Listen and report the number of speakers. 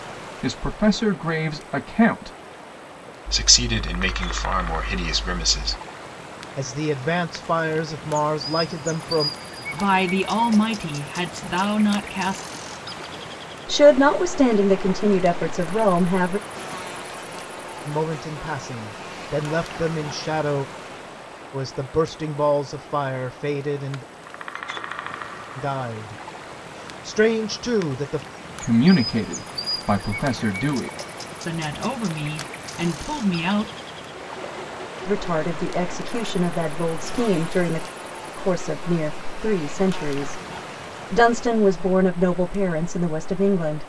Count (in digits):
5